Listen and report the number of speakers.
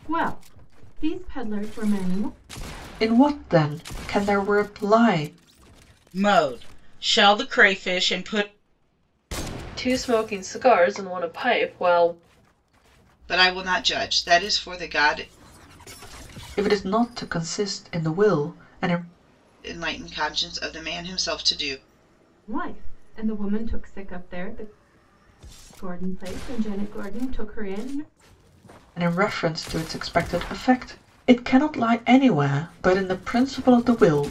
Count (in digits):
5